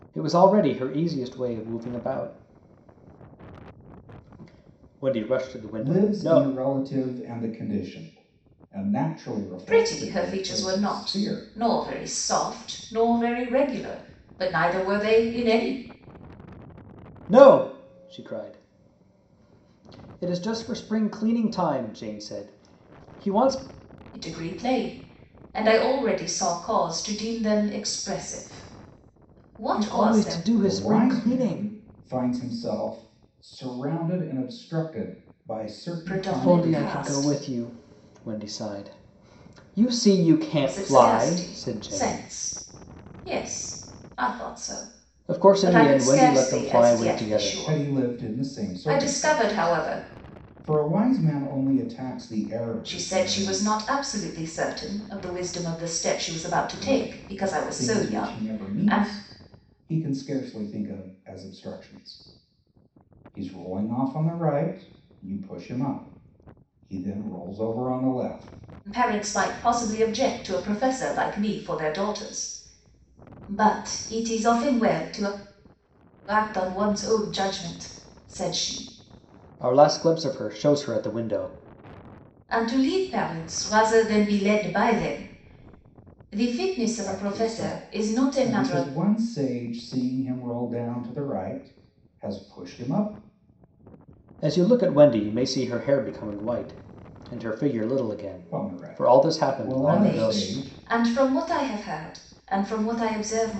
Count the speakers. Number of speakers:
three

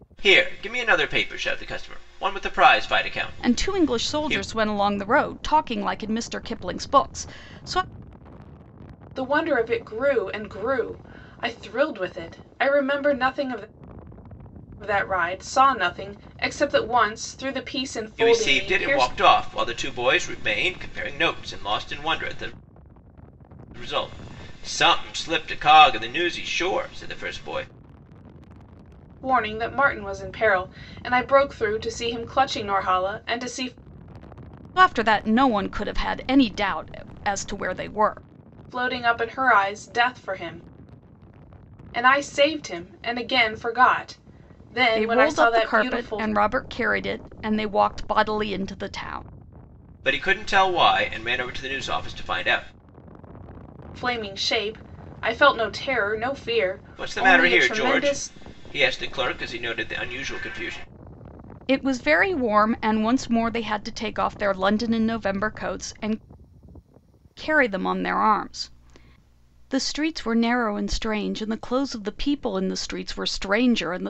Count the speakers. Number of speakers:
three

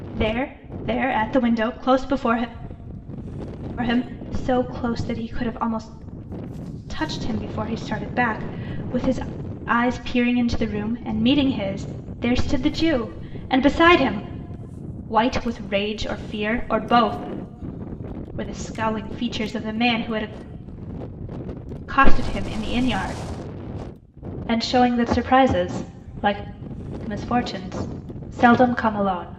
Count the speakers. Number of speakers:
one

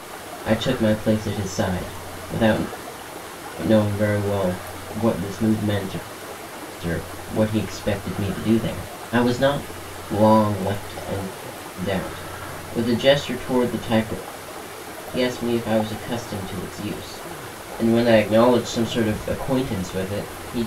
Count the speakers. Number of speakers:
one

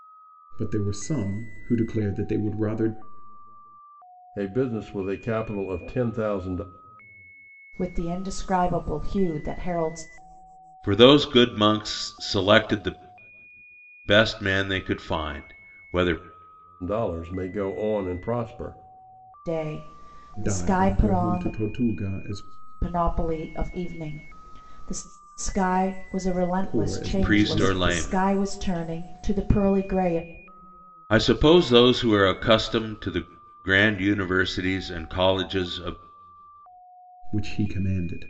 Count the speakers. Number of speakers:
four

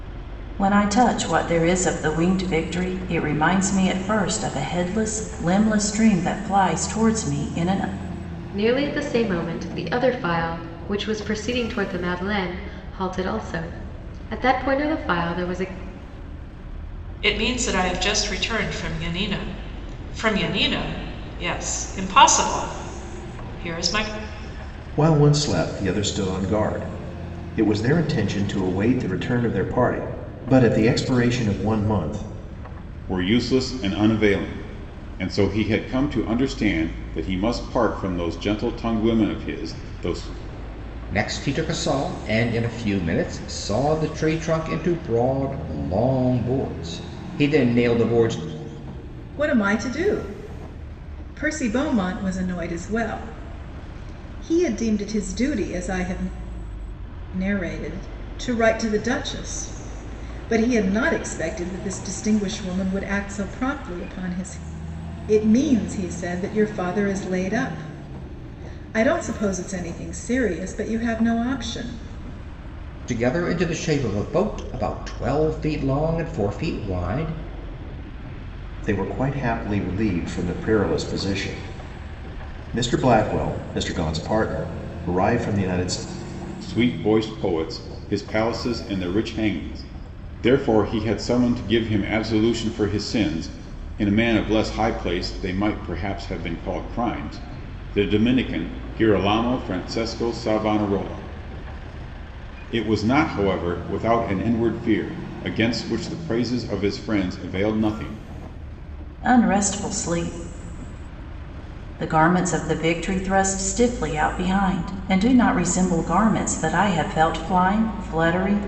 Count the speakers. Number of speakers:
seven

